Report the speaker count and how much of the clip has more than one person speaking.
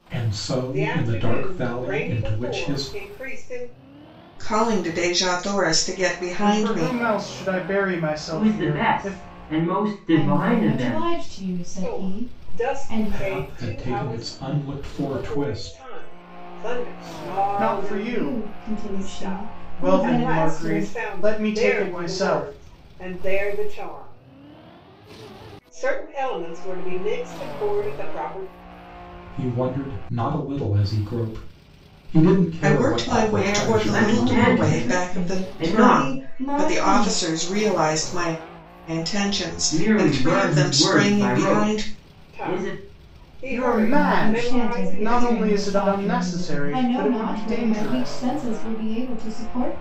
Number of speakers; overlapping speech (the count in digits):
6, about 51%